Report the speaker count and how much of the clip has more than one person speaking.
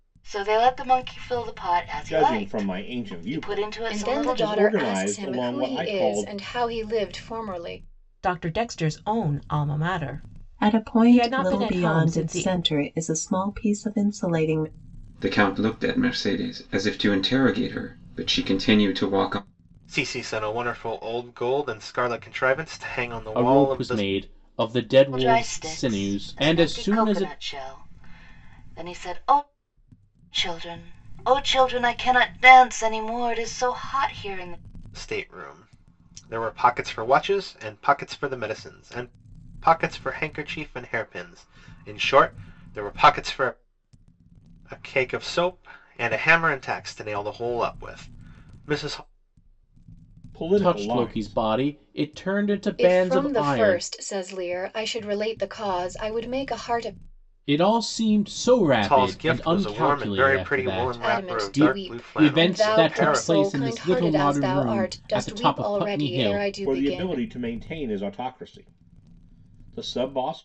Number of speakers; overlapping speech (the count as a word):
eight, about 28%